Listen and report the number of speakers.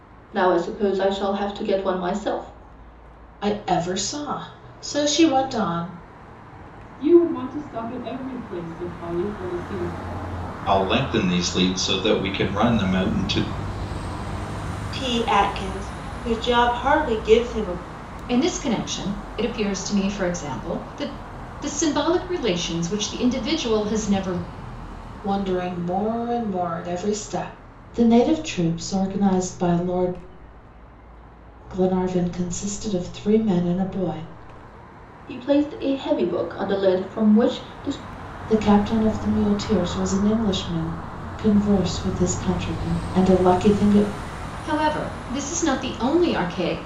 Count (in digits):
6